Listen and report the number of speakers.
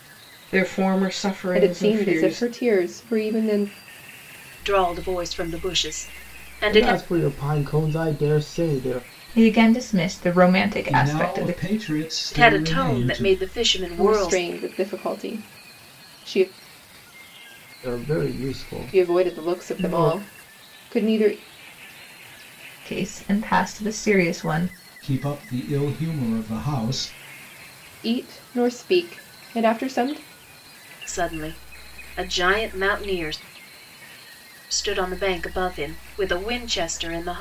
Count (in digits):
6